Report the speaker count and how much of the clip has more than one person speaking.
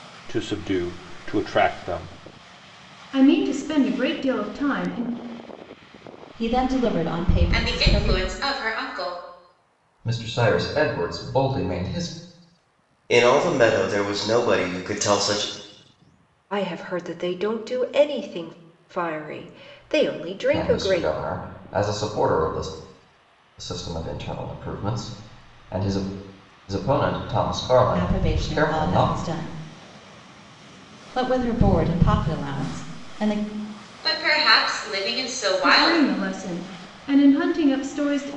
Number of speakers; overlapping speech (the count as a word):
seven, about 9%